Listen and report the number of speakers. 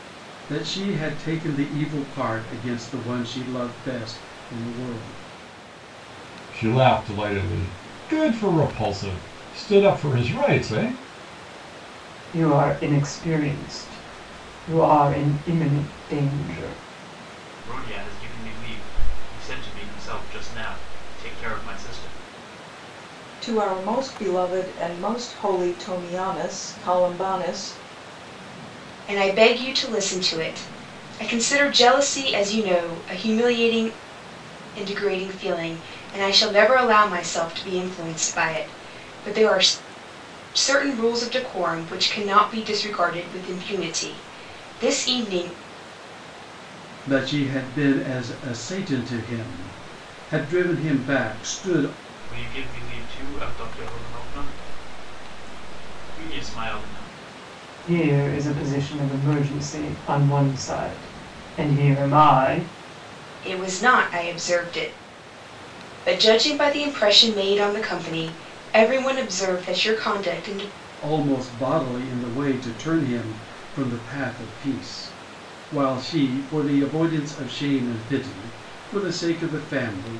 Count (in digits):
6